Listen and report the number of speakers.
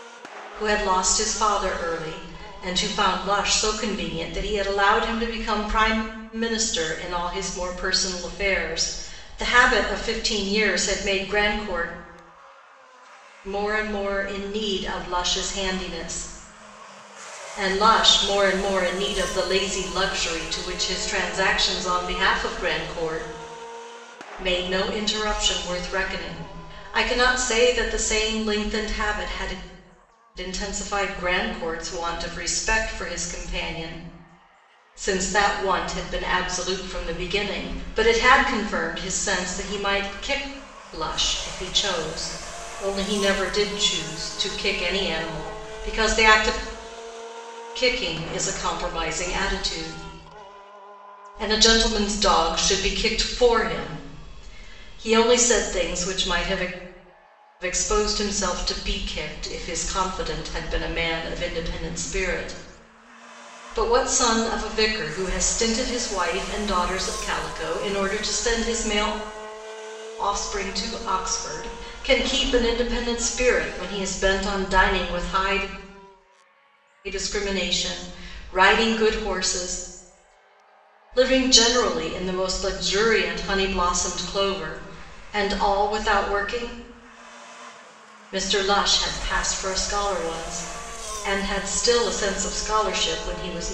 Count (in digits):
1